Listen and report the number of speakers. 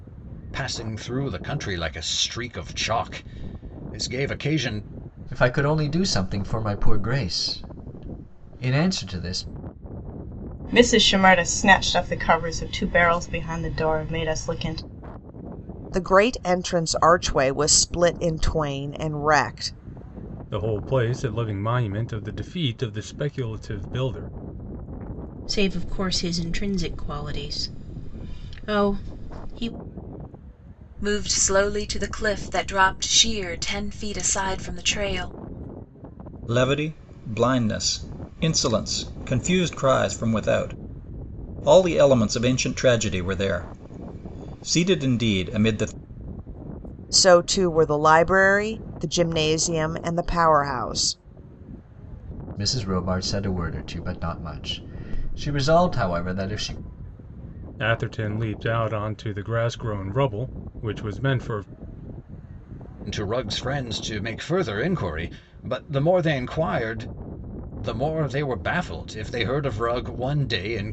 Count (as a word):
eight